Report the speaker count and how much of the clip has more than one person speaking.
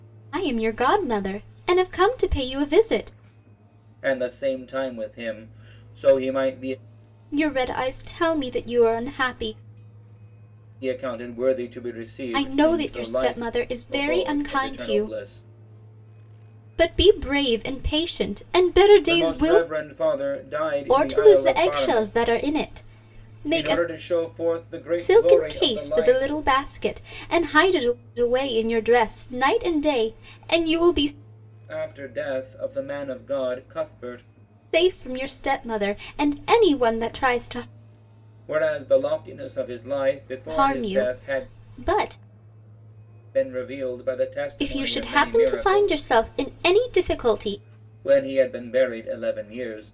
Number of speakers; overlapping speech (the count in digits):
2, about 17%